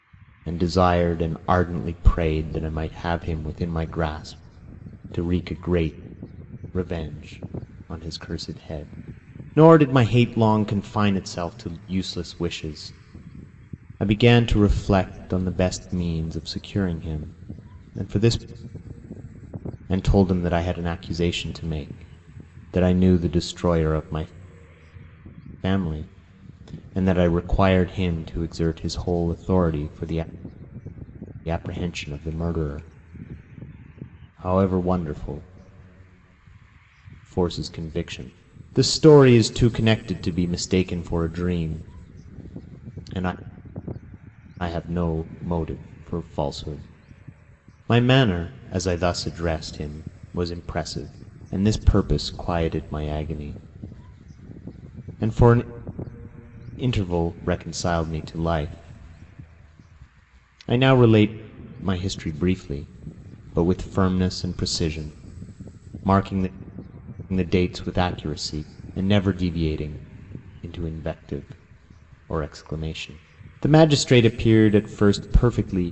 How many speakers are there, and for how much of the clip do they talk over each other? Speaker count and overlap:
1, no overlap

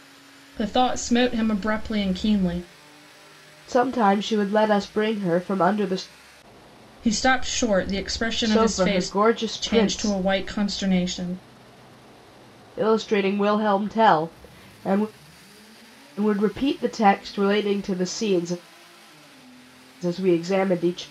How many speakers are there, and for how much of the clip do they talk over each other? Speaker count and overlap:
2, about 6%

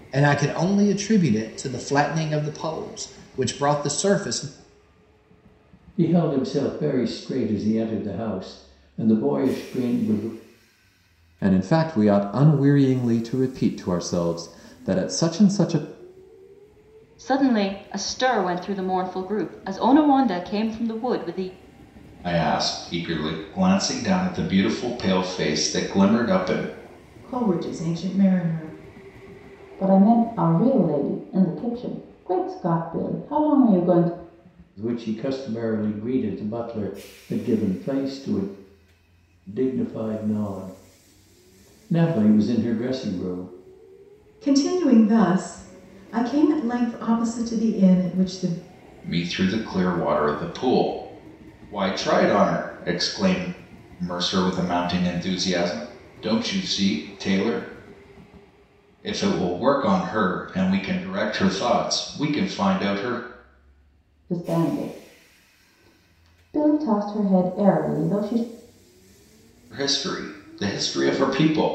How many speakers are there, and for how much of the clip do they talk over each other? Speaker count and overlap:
7, no overlap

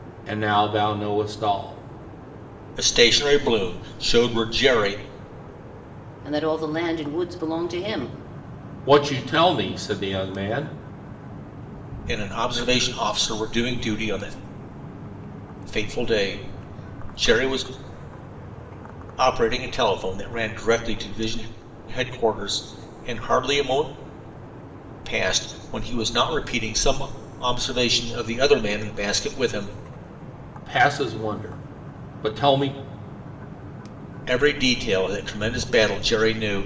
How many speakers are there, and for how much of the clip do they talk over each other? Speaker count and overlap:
3, no overlap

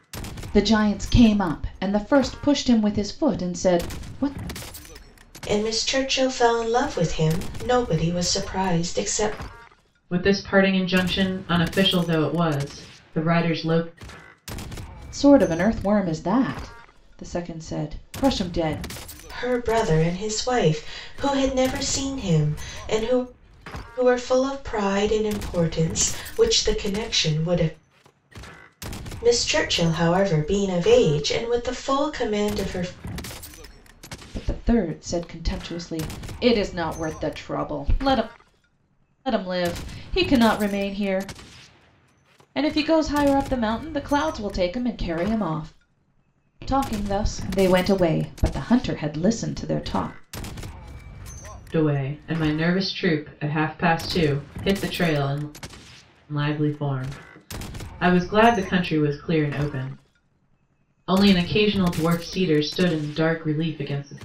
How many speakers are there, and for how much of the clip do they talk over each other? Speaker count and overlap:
3, no overlap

